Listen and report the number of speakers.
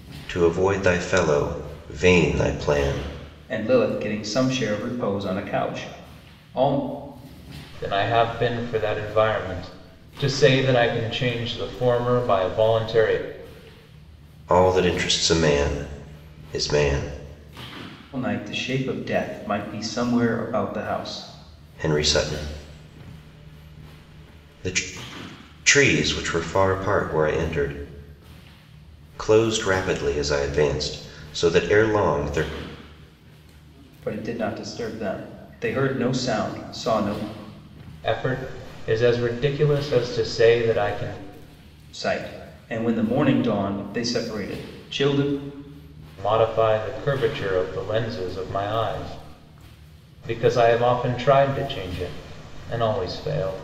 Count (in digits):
3